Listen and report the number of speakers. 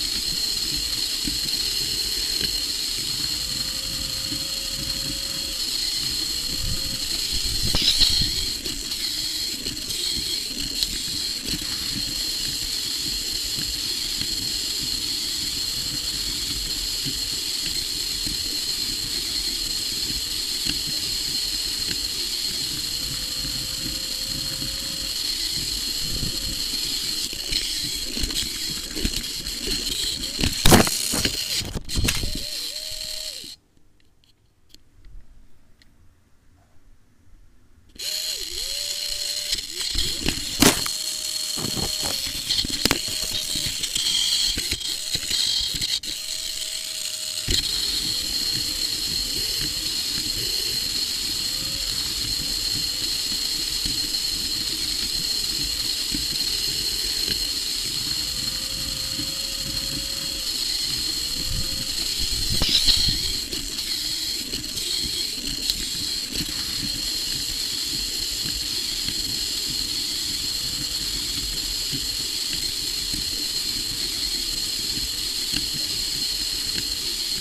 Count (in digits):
0